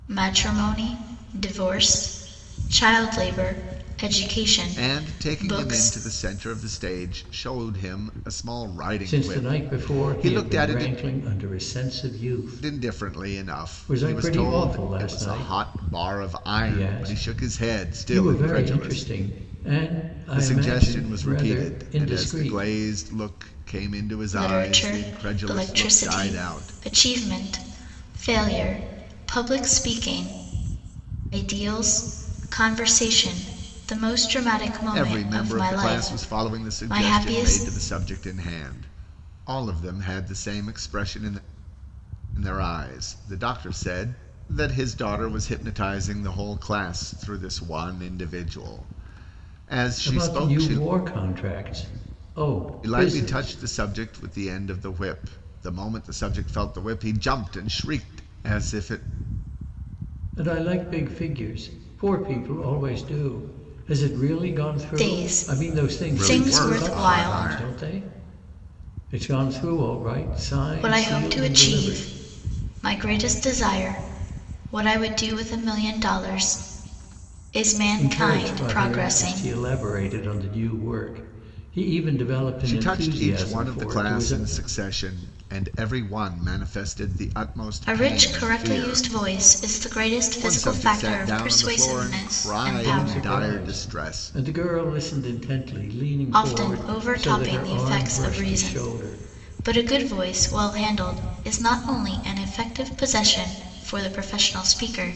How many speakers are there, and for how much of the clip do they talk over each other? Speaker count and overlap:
3, about 32%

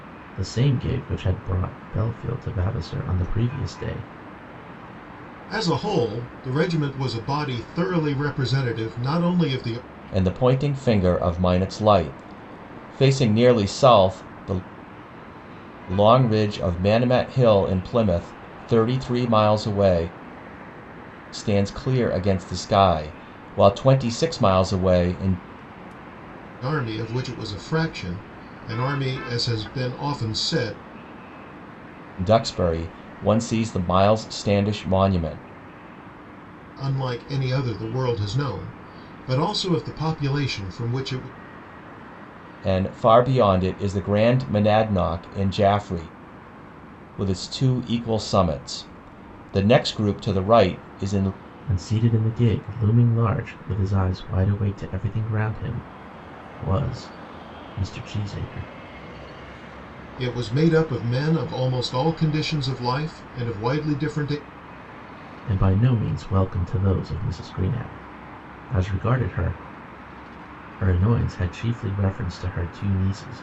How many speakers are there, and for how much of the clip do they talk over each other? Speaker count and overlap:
3, no overlap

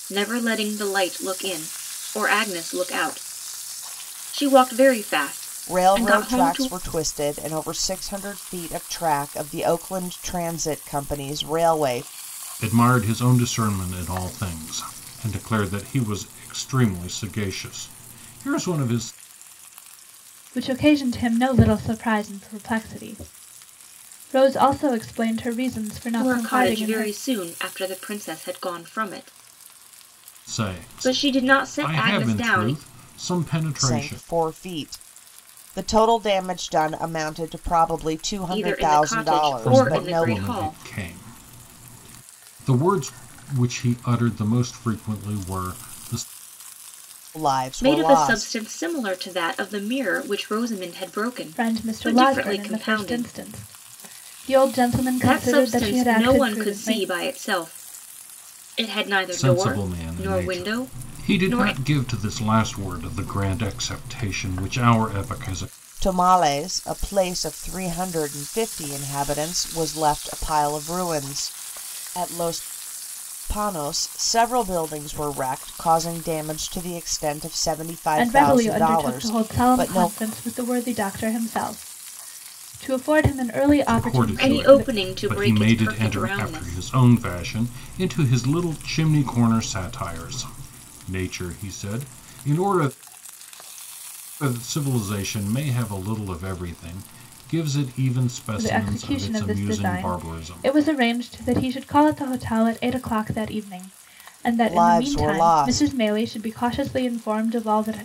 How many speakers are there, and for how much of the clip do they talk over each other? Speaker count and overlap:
4, about 21%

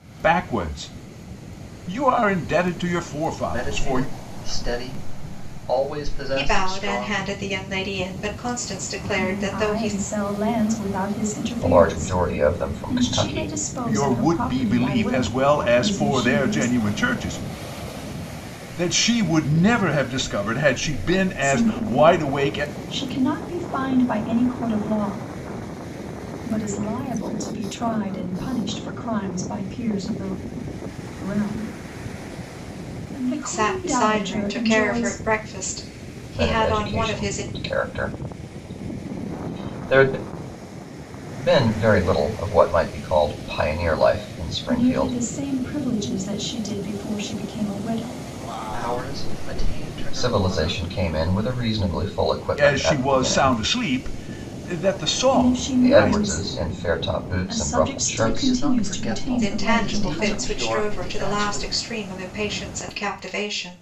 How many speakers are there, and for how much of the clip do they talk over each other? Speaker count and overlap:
5, about 30%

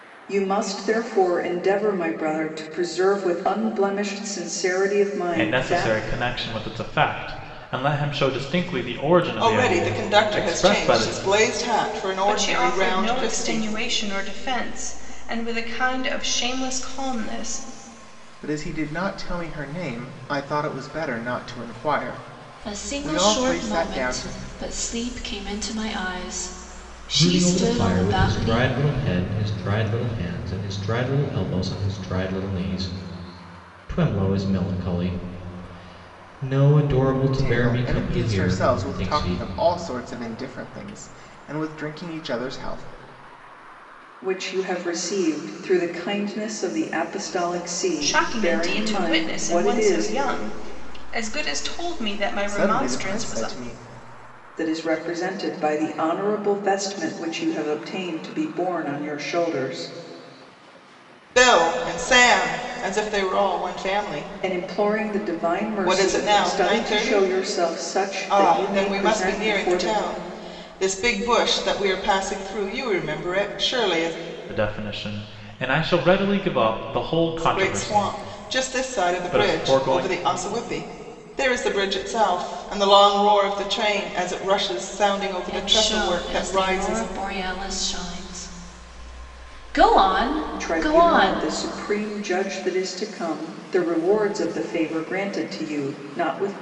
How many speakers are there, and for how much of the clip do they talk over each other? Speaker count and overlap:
7, about 23%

